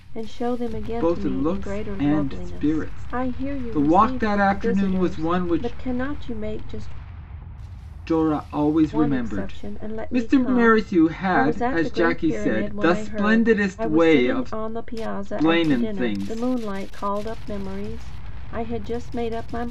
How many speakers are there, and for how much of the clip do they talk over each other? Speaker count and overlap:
two, about 53%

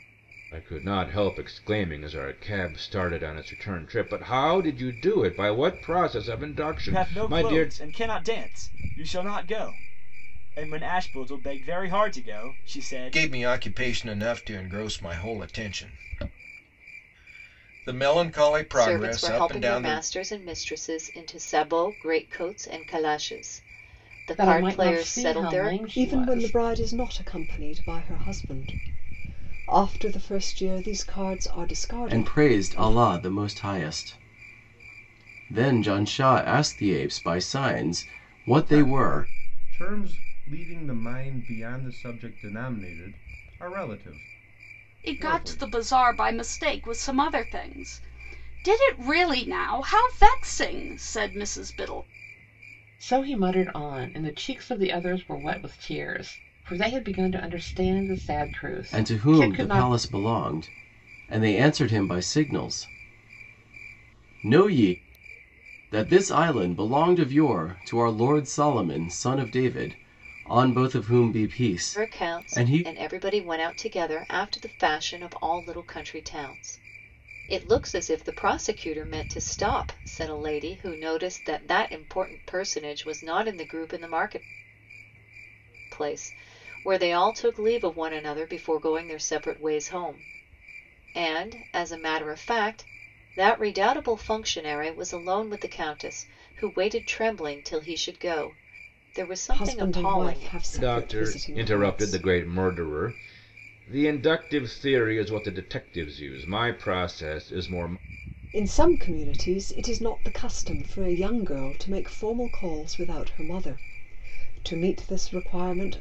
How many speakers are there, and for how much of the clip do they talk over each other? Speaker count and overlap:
nine, about 10%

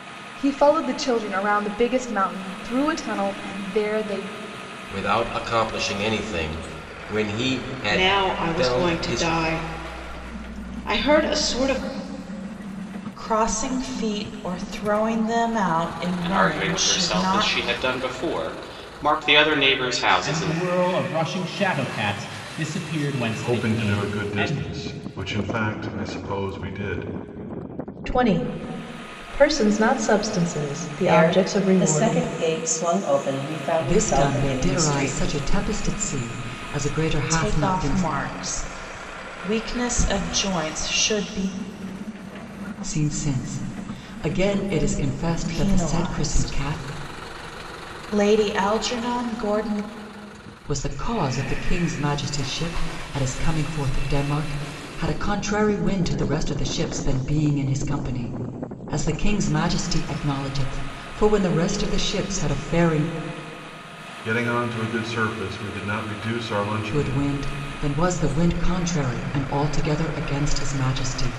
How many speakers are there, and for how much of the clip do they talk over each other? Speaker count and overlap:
ten, about 14%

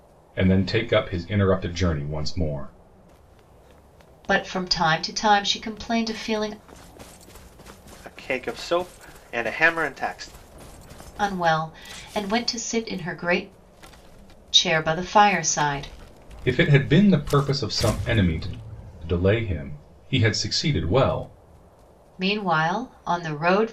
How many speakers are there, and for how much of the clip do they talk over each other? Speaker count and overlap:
three, no overlap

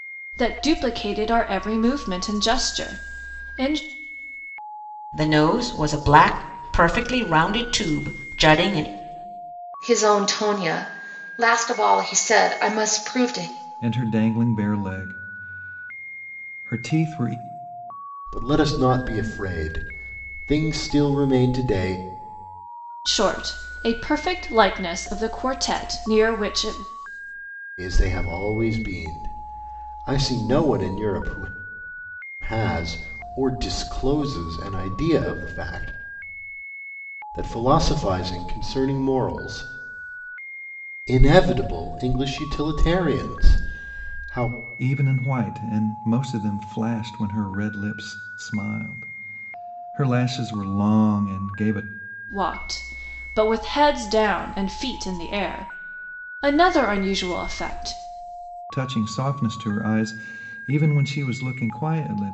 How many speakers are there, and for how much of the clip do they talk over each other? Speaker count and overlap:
five, no overlap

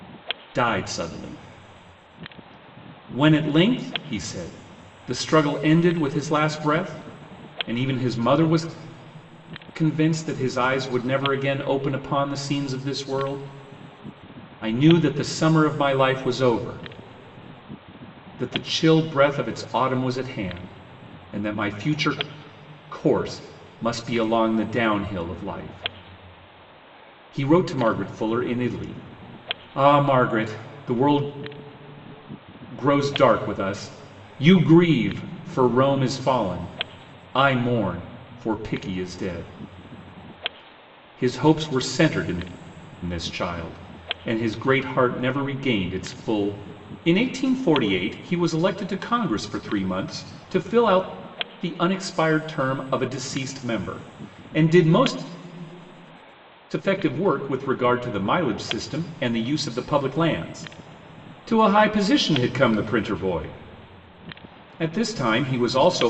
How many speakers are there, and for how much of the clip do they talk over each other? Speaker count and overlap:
one, no overlap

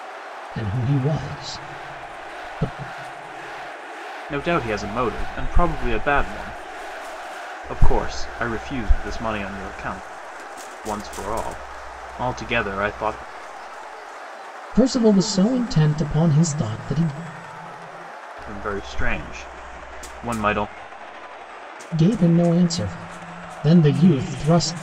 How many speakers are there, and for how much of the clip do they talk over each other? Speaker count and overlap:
two, no overlap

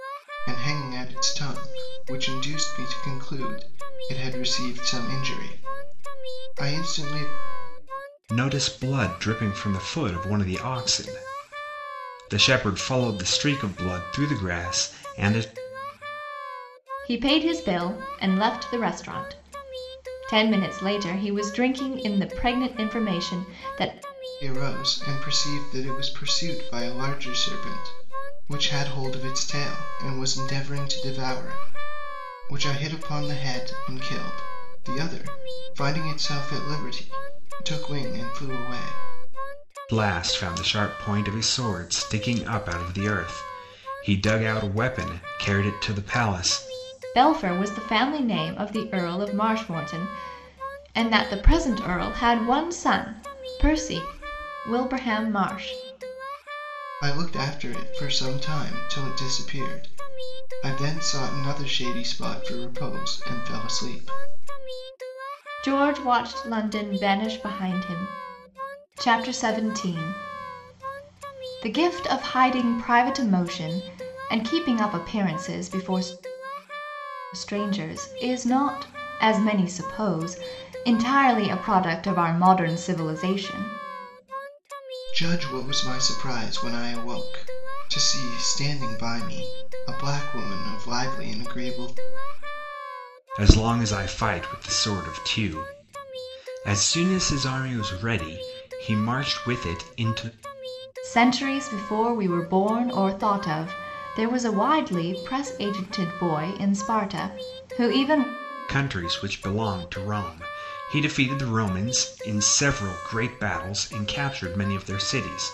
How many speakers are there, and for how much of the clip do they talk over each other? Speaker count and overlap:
three, no overlap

